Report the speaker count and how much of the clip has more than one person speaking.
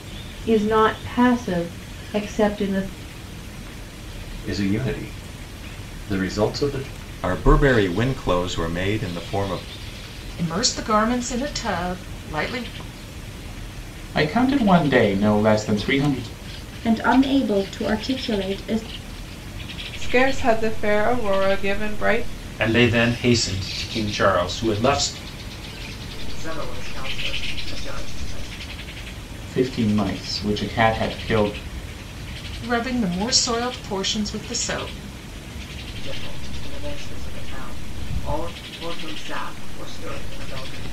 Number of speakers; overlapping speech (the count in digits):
9, no overlap